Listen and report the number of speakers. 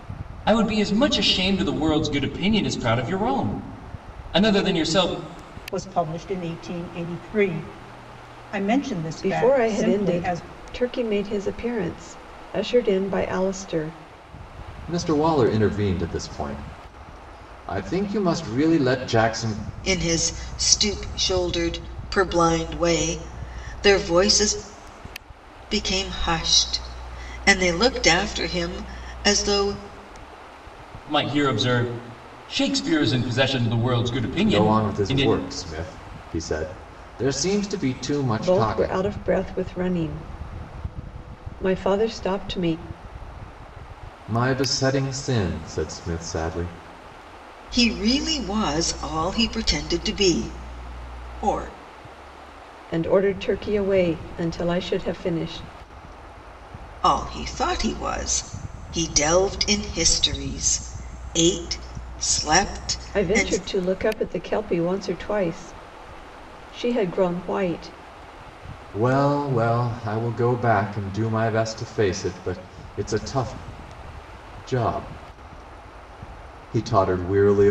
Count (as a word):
five